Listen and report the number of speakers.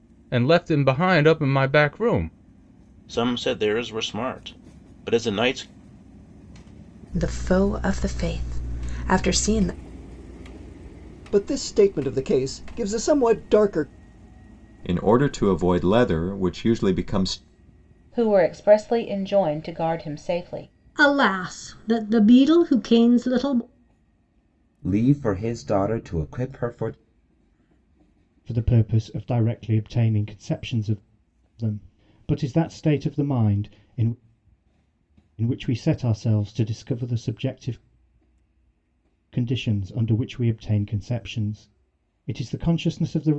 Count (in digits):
9